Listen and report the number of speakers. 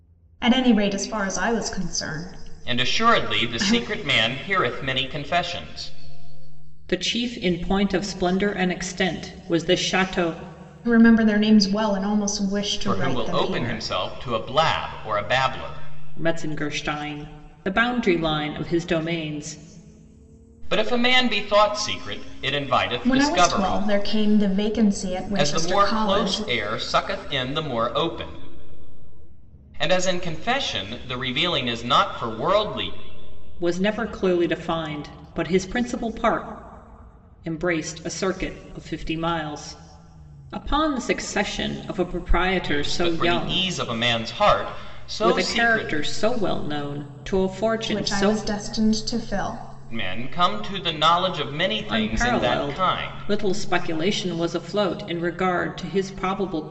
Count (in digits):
3